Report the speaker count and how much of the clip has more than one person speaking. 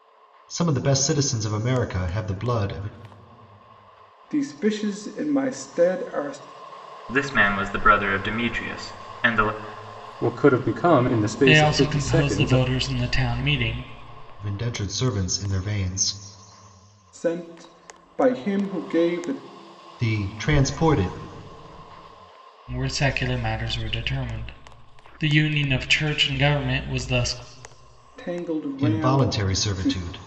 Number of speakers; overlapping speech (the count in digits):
5, about 8%